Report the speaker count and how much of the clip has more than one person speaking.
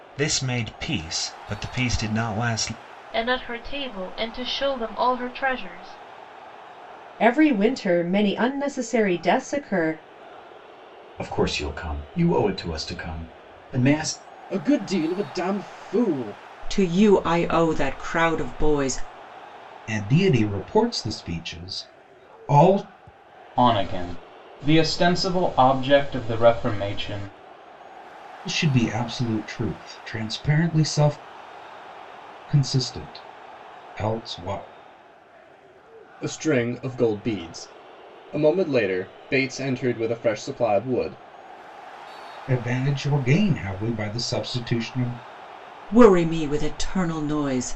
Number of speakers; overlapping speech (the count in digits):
8, no overlap